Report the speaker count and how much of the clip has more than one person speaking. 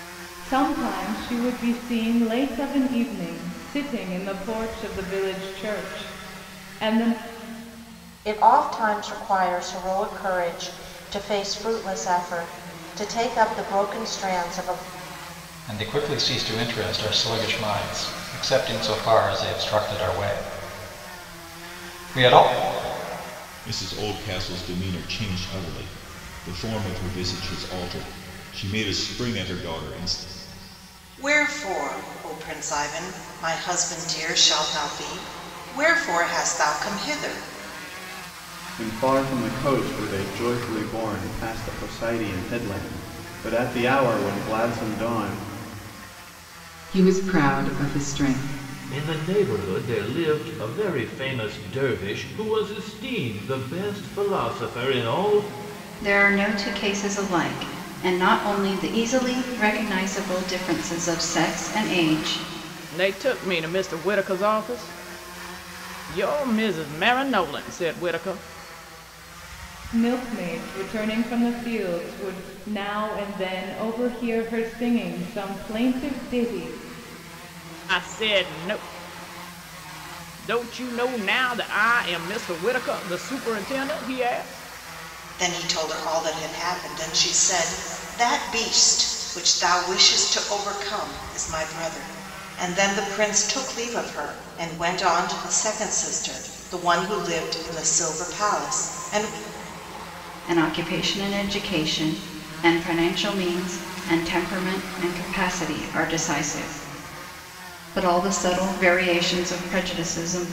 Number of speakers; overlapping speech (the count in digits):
10, no overlap